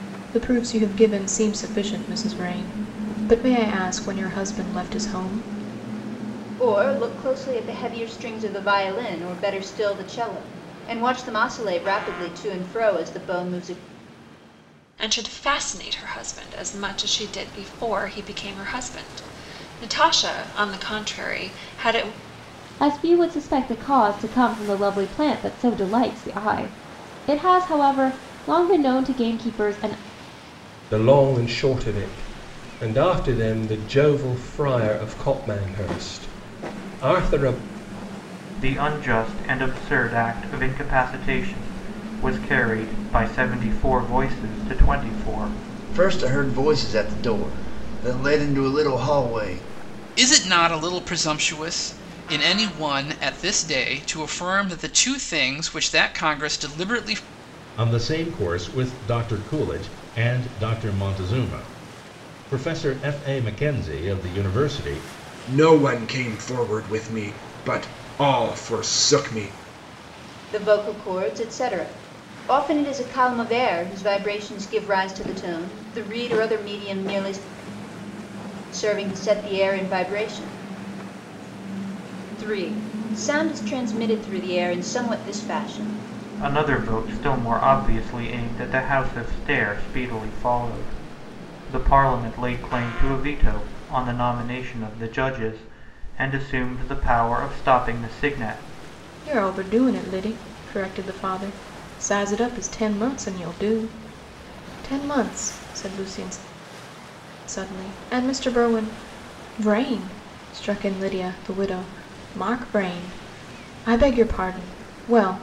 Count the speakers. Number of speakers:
10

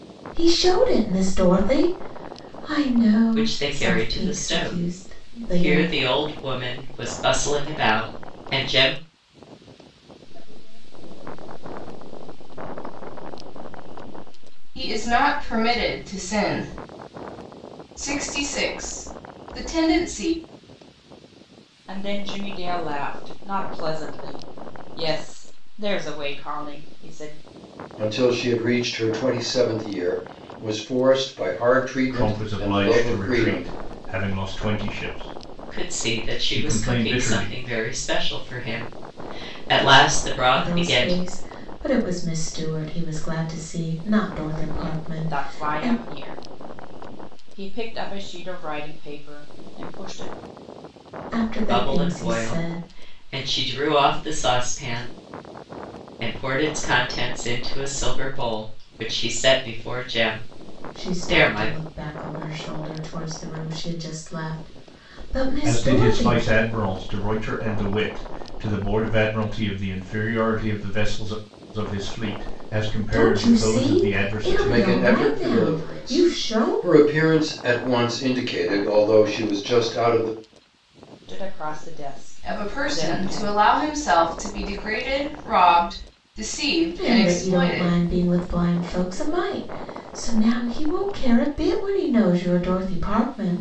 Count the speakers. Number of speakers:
7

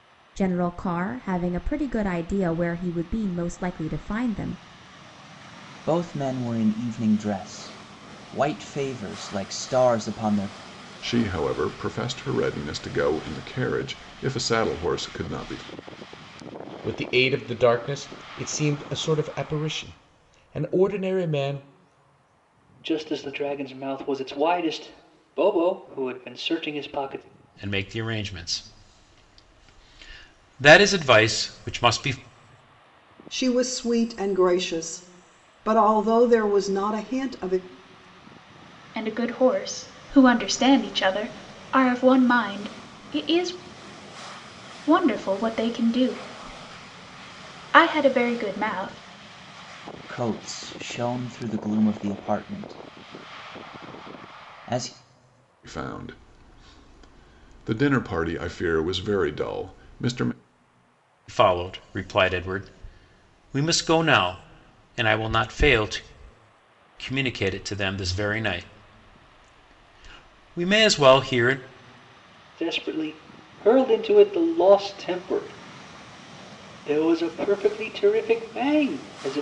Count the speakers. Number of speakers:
8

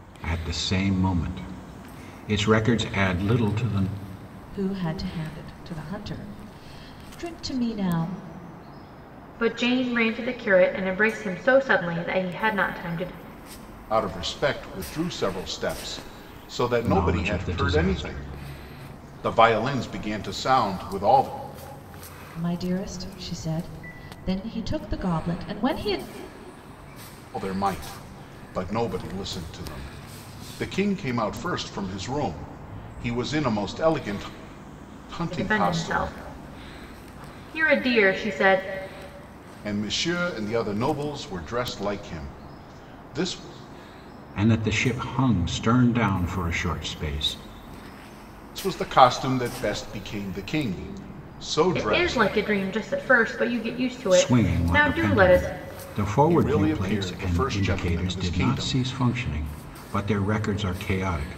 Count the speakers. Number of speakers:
4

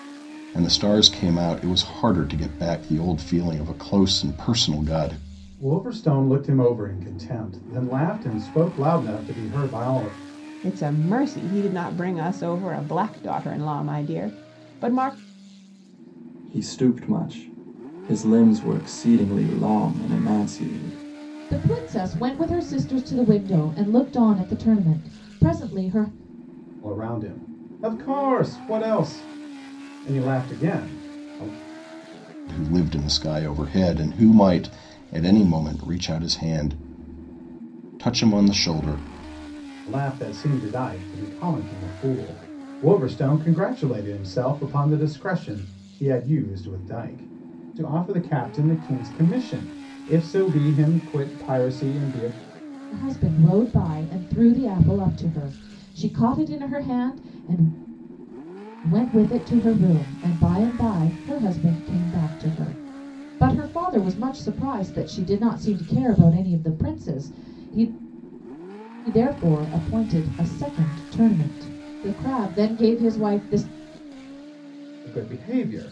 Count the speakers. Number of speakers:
5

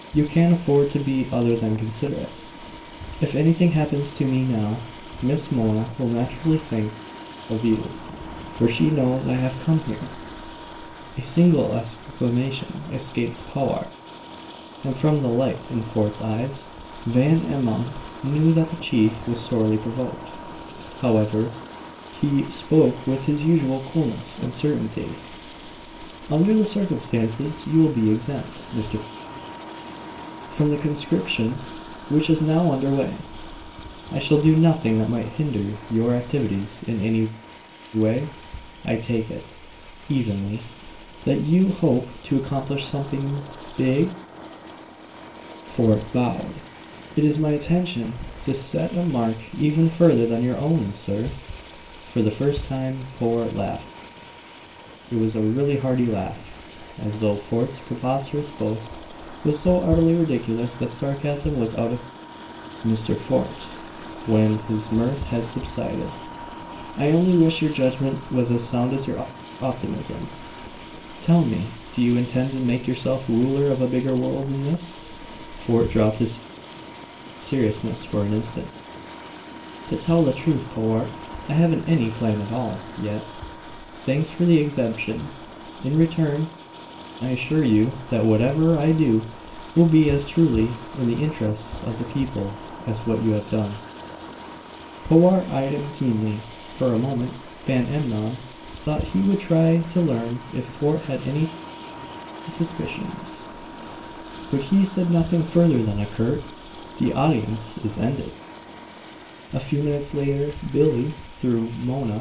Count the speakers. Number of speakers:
1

